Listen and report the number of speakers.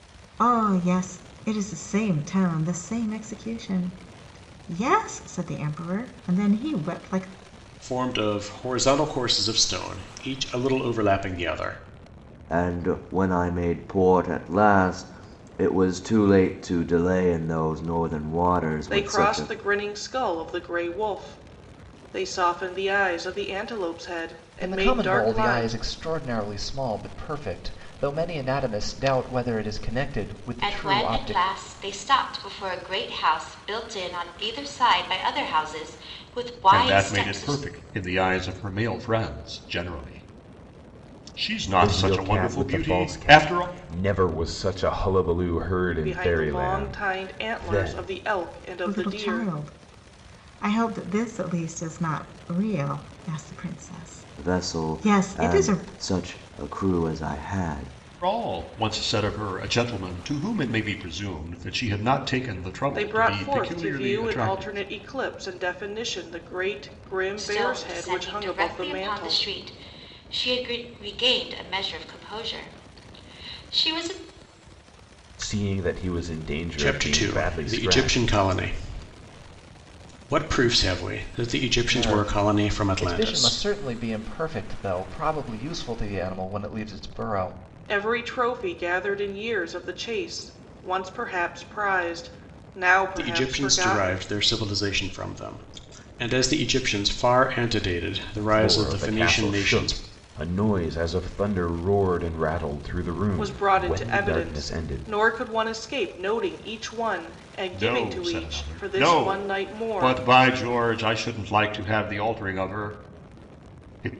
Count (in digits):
8